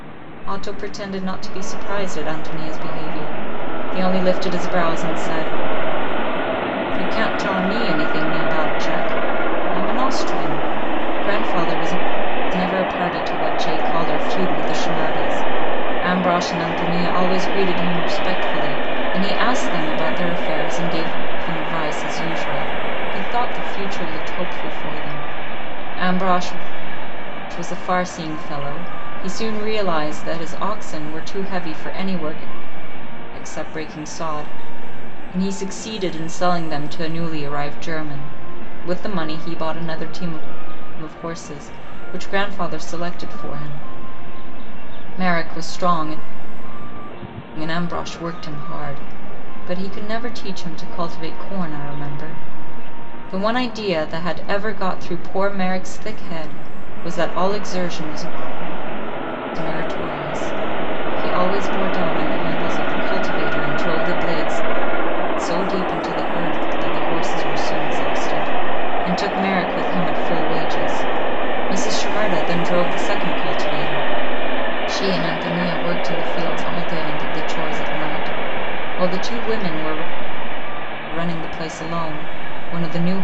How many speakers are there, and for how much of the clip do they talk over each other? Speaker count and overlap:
1, no overlap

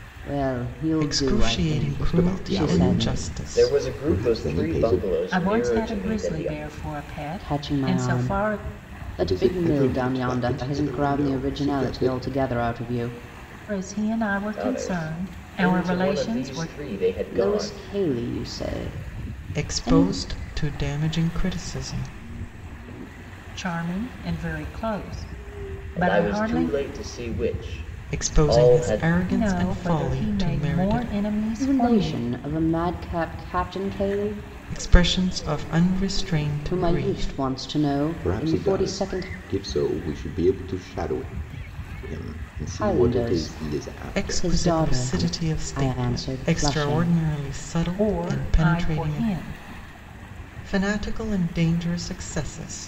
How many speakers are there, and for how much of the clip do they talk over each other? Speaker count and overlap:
5, about 47%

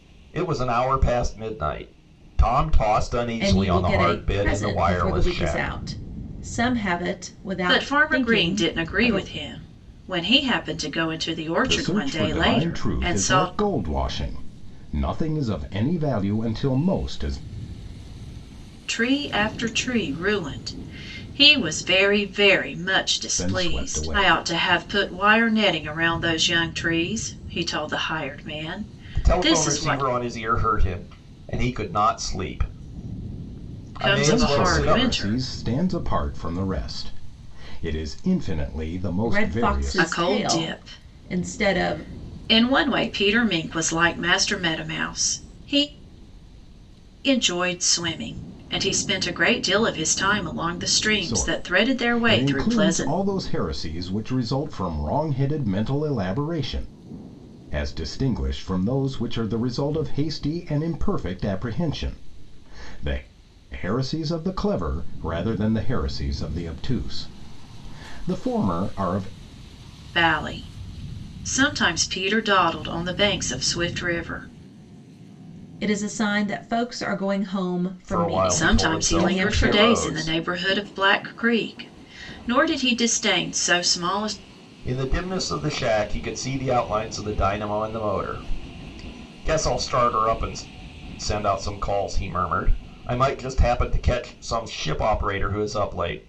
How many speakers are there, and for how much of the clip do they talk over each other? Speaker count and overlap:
4, about 17%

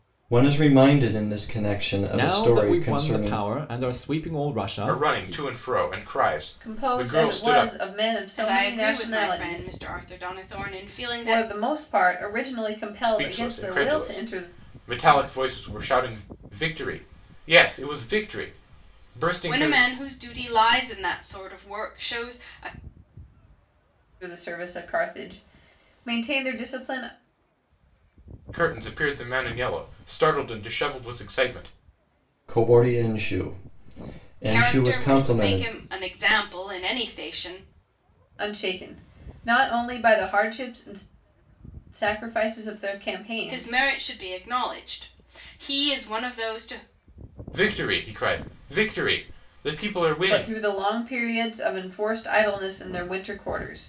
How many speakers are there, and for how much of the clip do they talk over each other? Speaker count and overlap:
5, about 17%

